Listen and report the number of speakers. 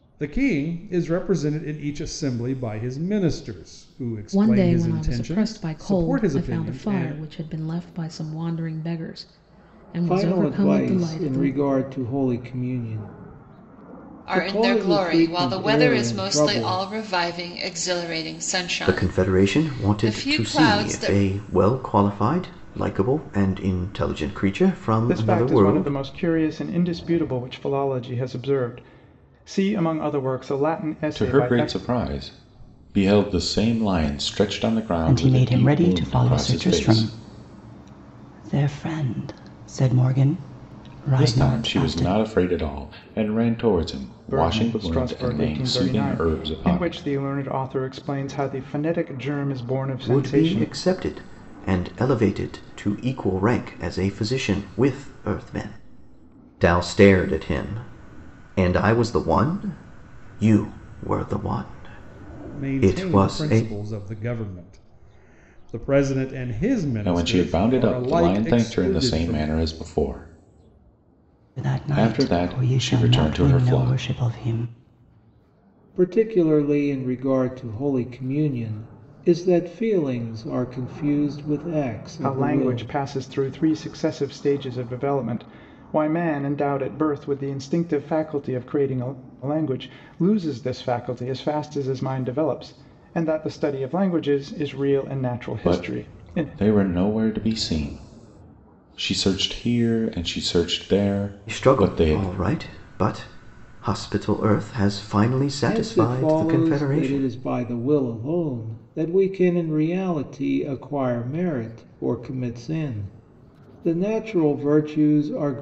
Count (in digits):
8